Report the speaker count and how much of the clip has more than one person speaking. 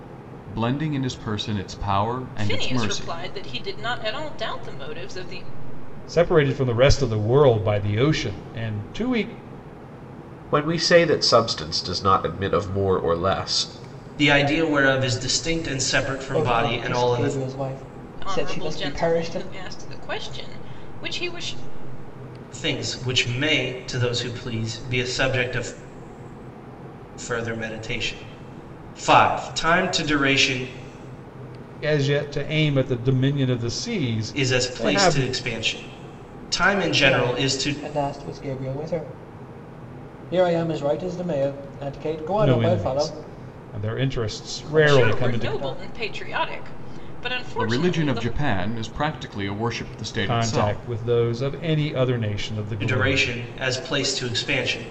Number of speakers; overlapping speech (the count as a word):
six, about 17%